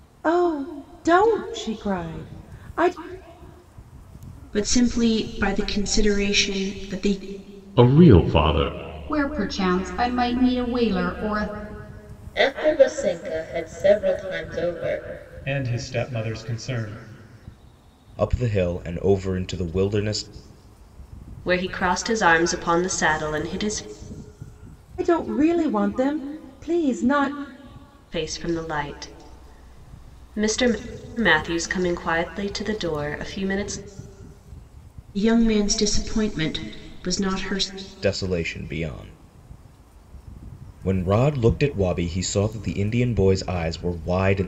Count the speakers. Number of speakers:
8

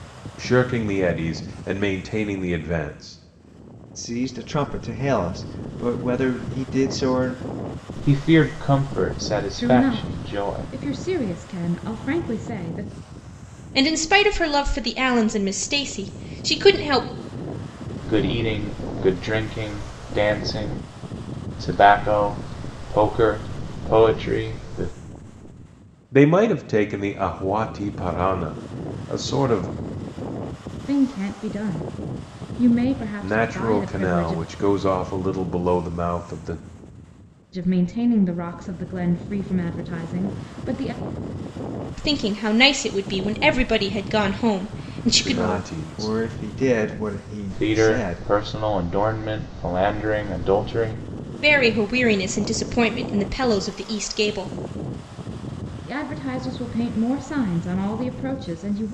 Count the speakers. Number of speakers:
5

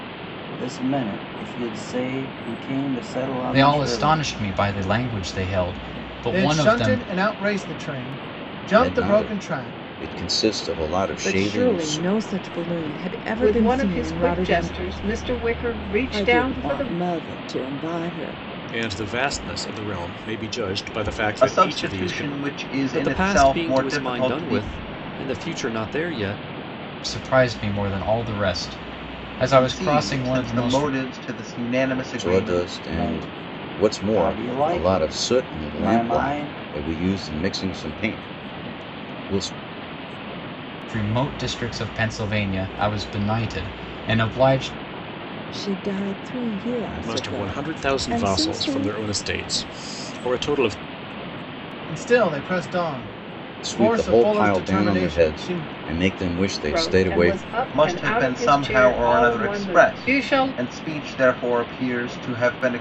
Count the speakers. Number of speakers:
10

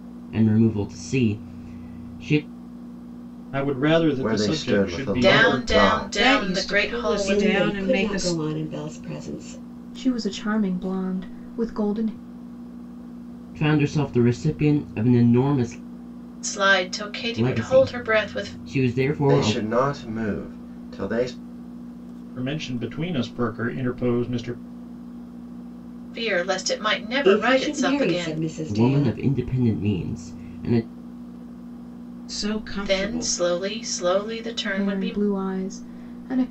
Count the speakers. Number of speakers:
7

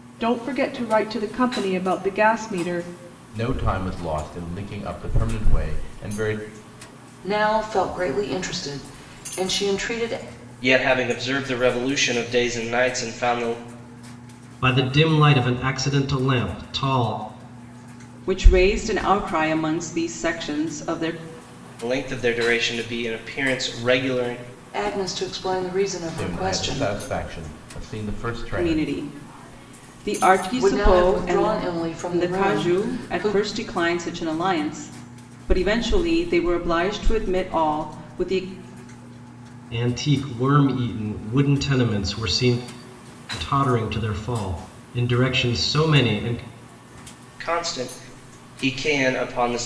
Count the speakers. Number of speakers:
6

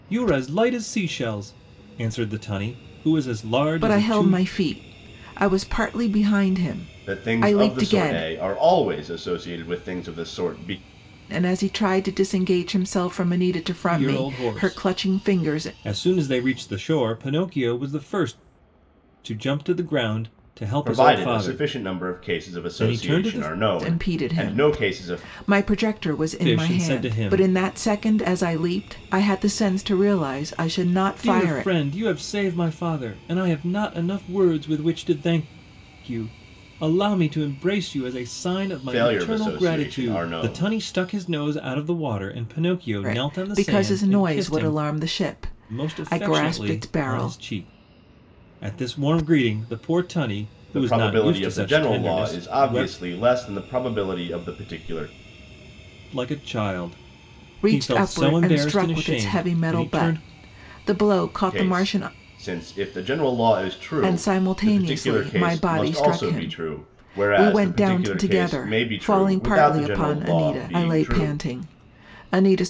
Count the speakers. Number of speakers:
3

